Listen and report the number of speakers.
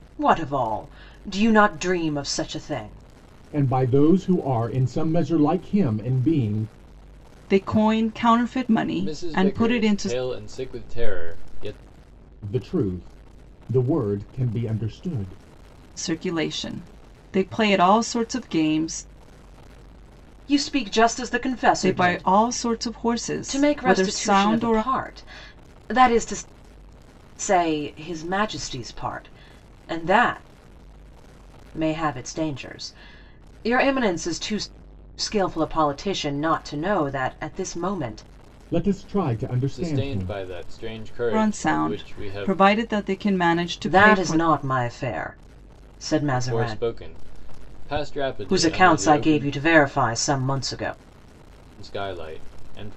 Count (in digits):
4